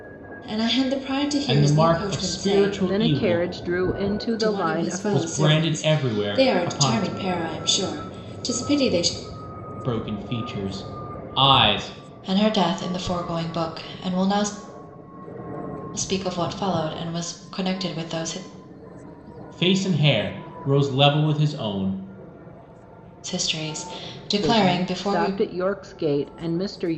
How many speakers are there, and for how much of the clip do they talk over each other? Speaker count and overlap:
three, about 22%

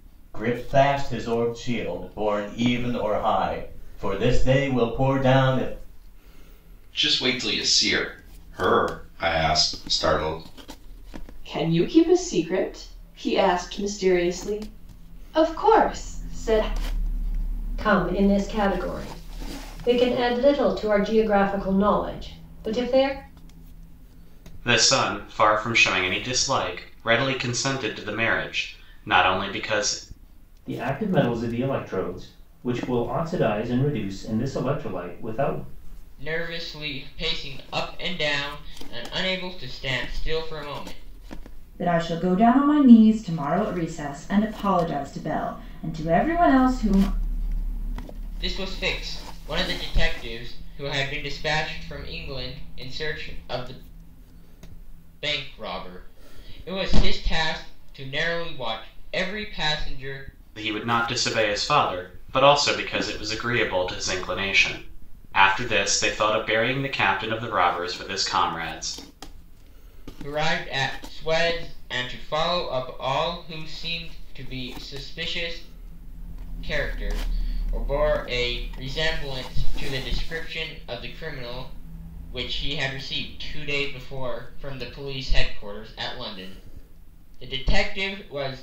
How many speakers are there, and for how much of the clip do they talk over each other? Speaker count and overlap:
eight, no overlap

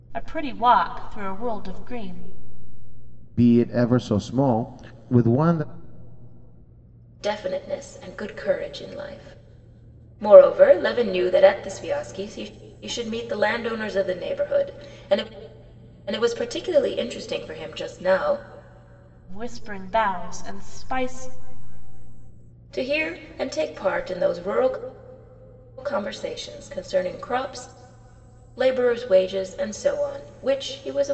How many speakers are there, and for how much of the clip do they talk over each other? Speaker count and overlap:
three, no overlap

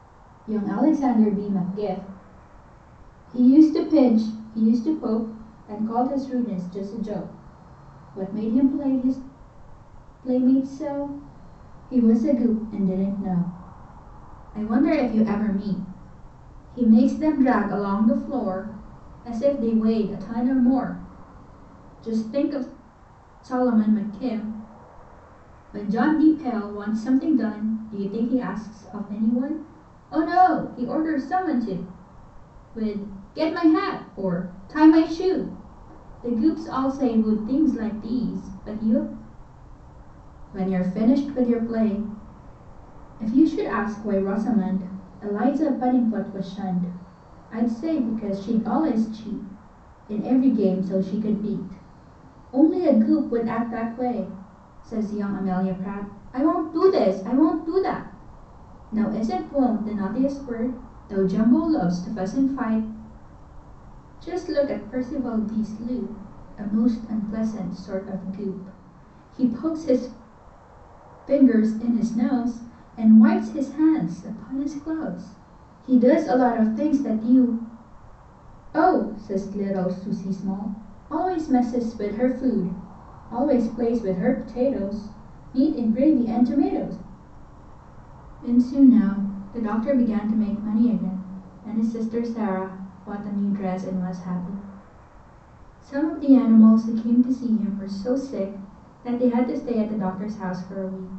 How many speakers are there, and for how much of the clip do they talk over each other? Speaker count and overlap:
one, no overlap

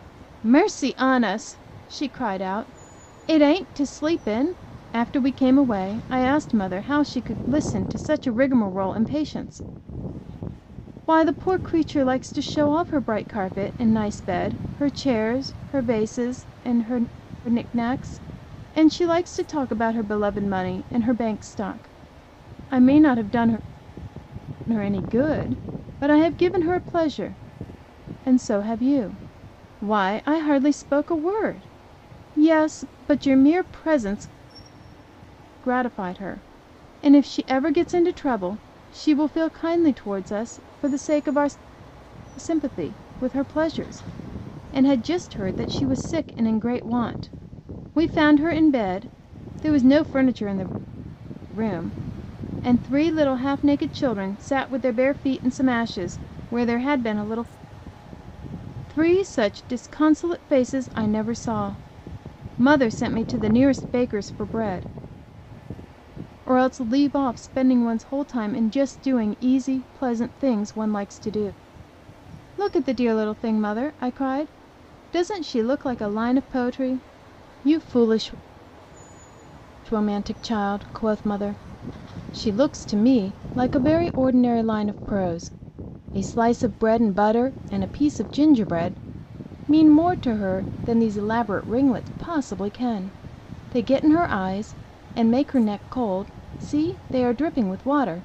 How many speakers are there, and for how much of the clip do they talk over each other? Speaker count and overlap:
one, no overlap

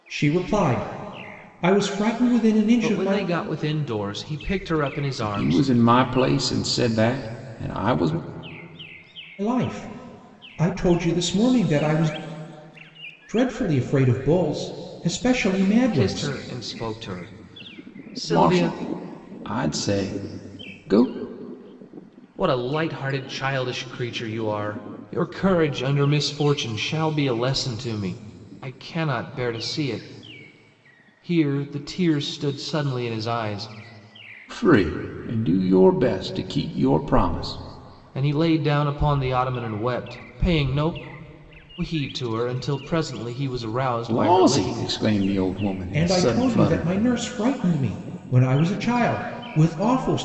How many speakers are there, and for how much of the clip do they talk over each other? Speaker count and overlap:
three, about 8%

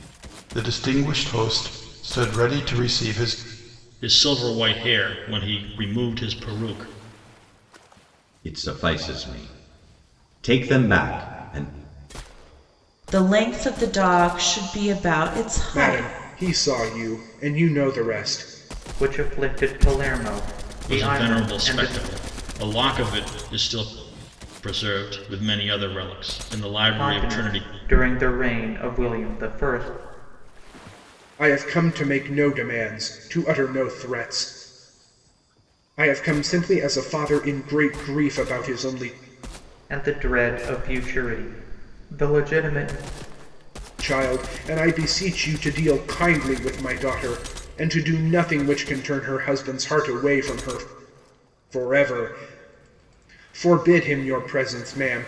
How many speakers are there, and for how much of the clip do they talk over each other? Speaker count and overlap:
six, about 5%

